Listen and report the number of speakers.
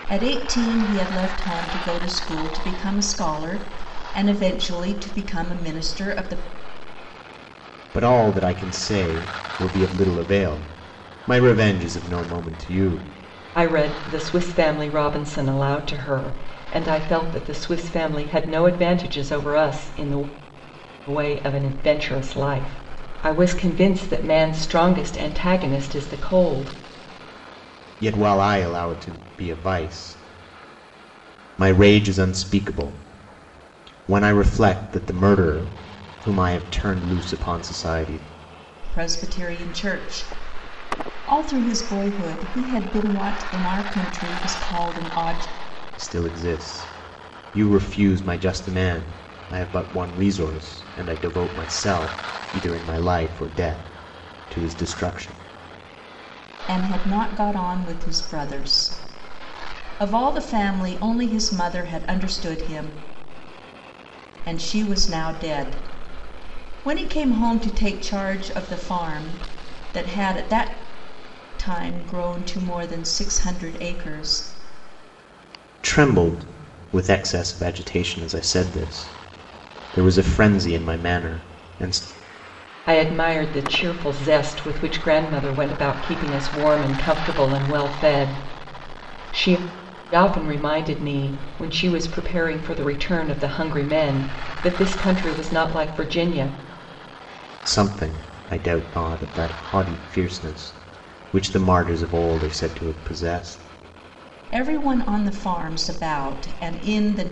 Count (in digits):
3